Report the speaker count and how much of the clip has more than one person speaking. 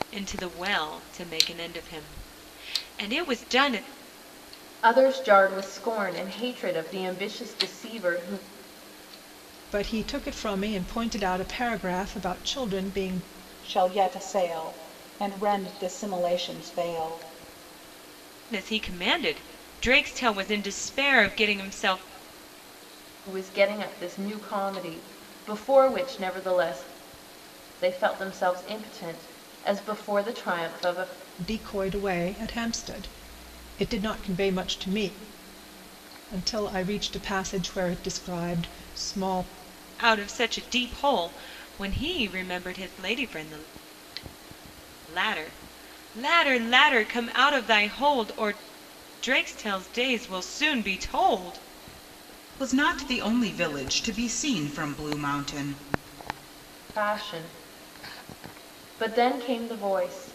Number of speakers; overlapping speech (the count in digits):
4, no overlap